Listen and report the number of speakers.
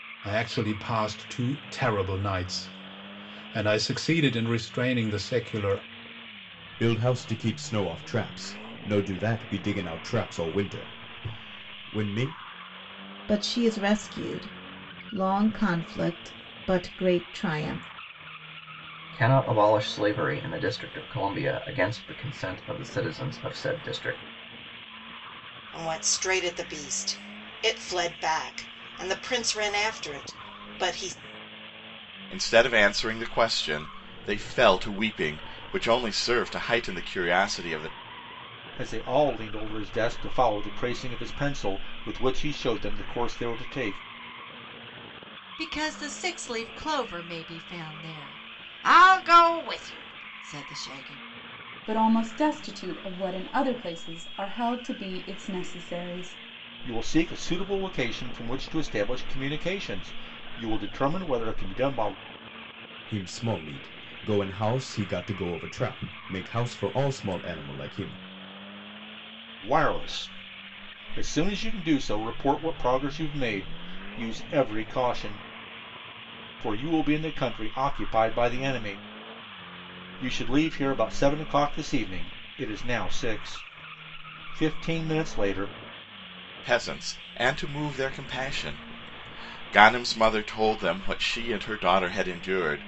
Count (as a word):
nine